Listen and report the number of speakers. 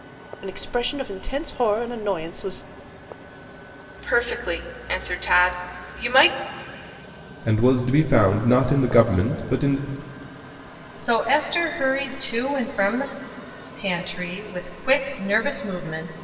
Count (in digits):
4